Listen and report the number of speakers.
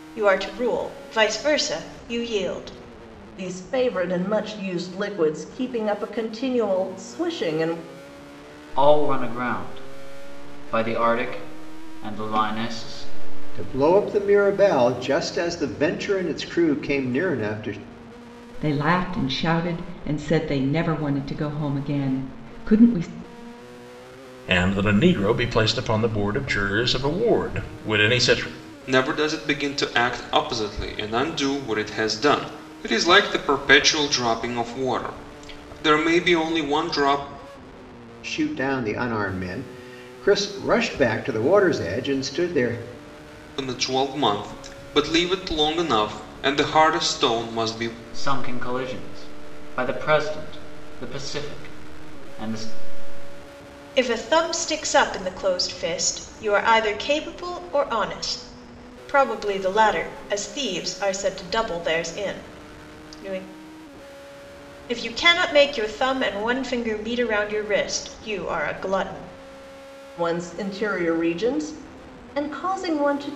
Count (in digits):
7